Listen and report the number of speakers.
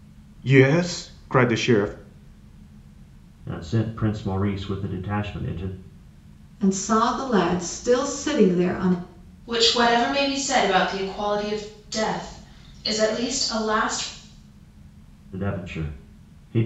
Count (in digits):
4